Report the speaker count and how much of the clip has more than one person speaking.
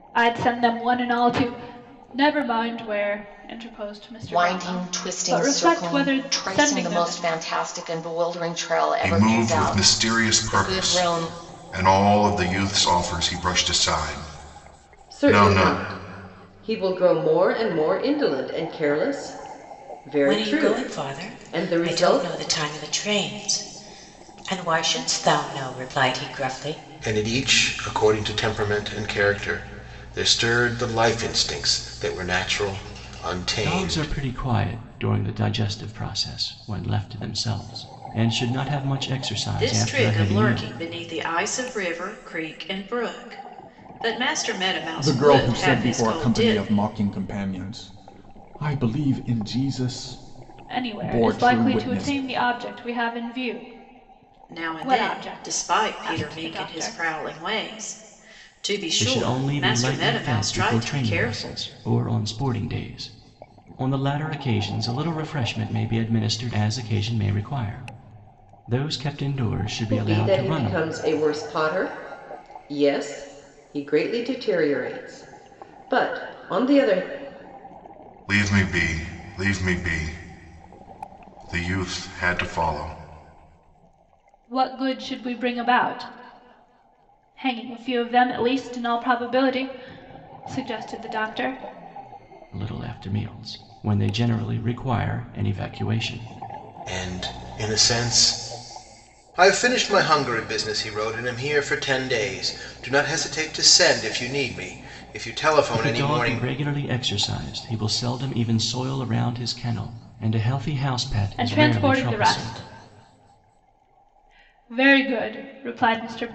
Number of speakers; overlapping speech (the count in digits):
9, about 18%